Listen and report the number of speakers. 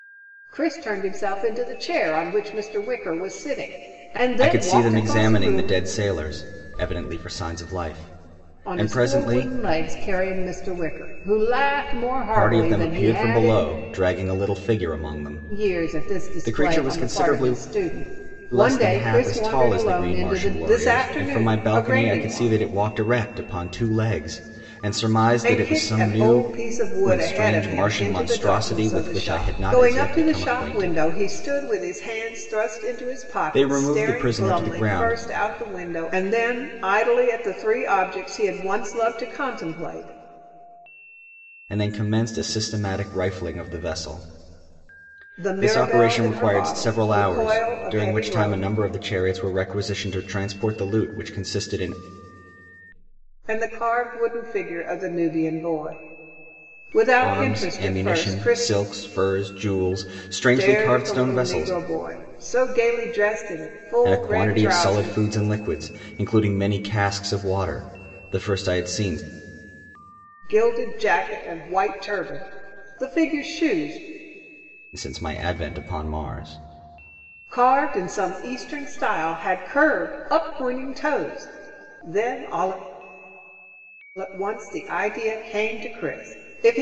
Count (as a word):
two